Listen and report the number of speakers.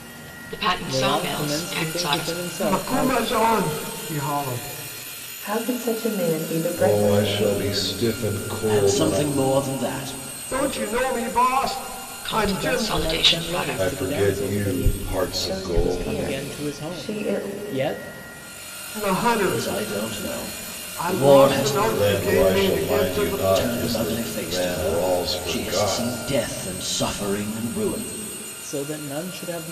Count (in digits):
6